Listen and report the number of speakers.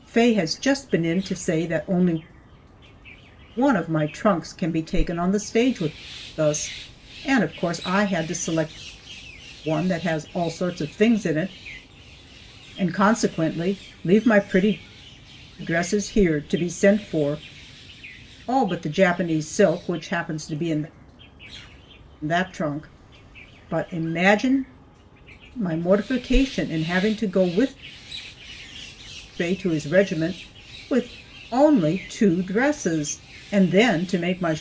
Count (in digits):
1